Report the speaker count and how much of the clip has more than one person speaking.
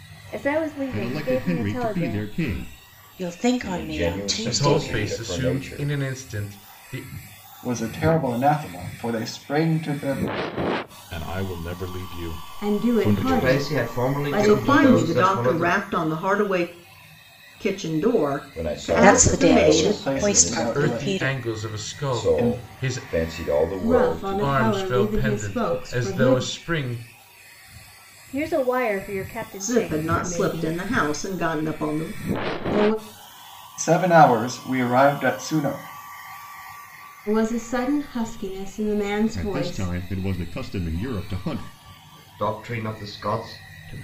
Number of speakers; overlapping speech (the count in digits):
10, about 39%